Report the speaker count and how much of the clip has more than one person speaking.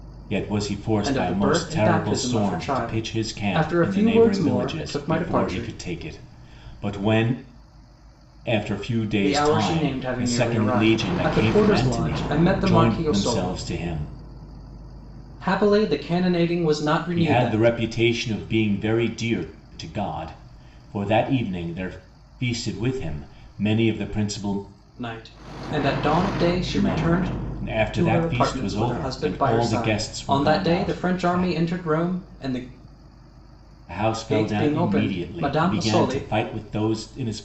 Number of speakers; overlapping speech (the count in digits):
2, about 41%